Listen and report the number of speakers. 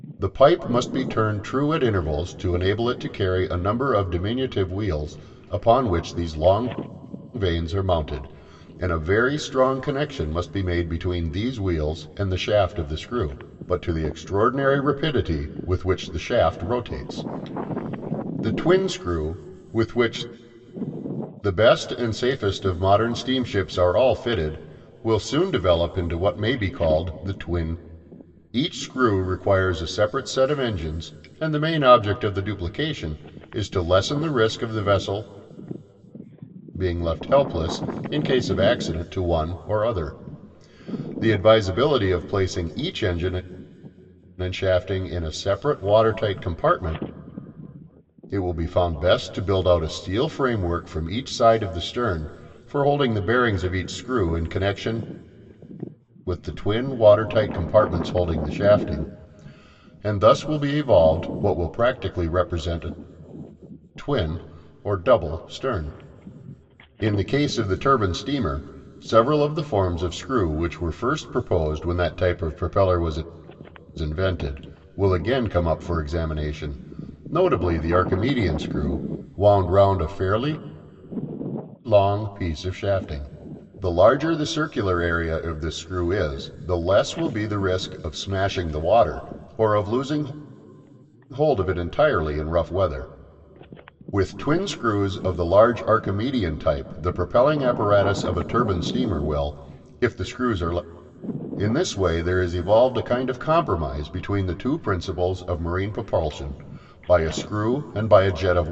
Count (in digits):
1